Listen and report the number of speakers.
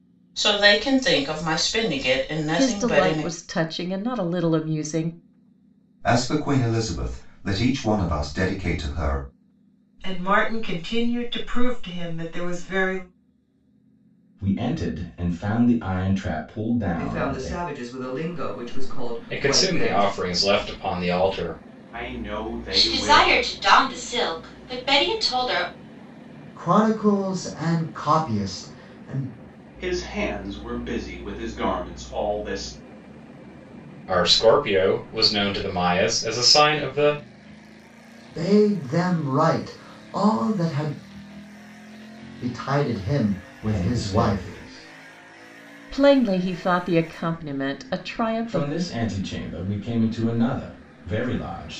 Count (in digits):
10